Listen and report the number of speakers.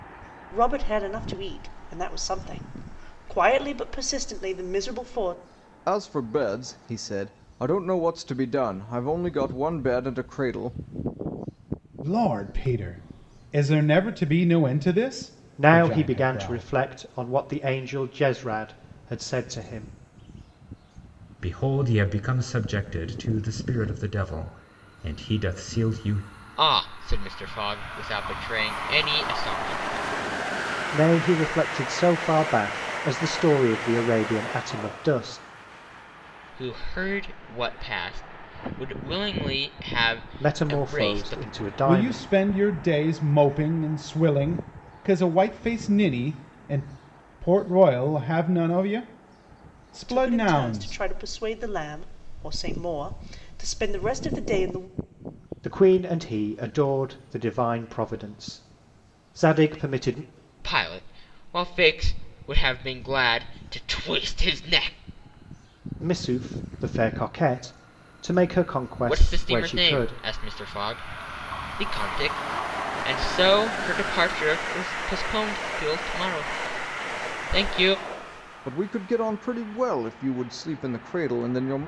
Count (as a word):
six